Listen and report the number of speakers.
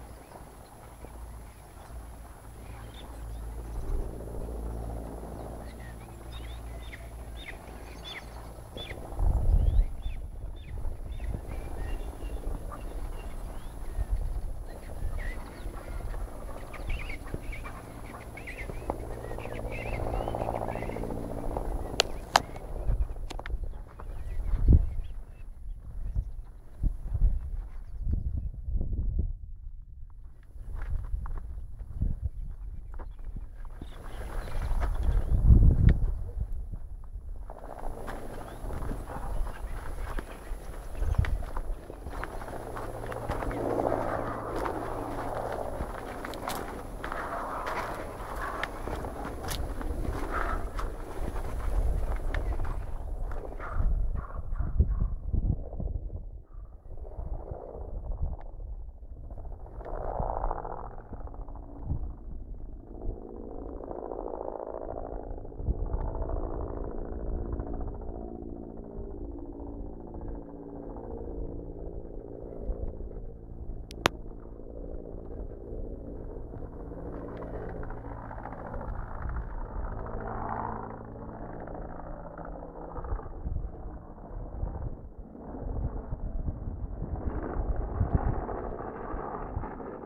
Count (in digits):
0